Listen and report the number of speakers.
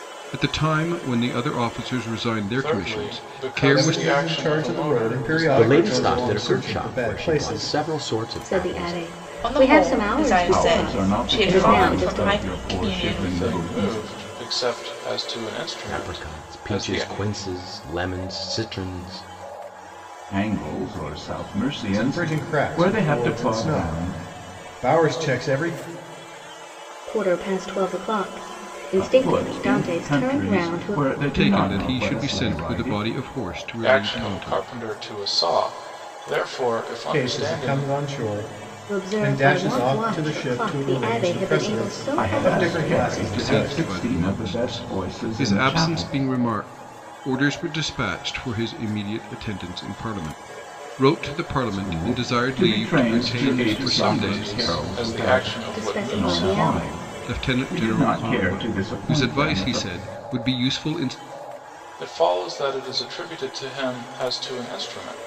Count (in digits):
7